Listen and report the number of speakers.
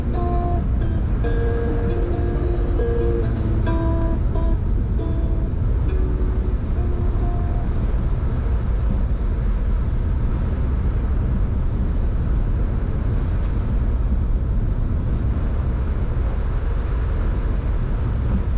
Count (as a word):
zero